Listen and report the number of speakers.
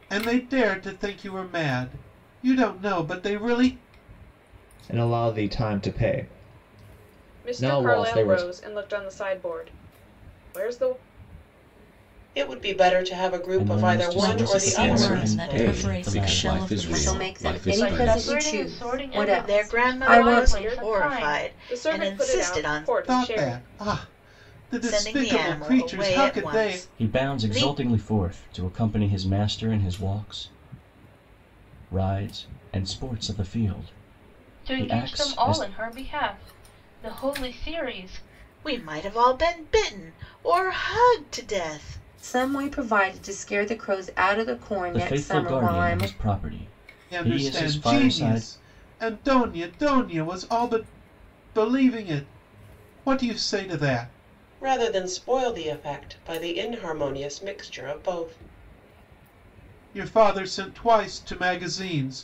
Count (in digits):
10